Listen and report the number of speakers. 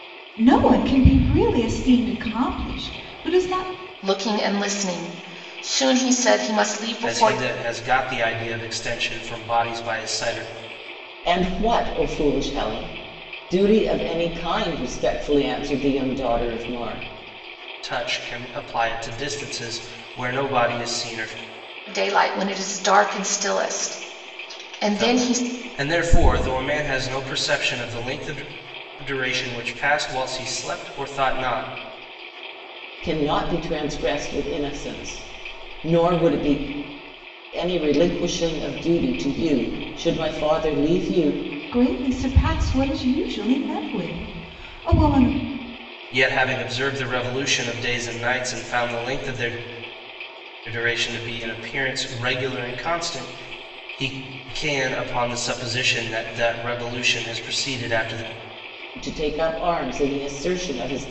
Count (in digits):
4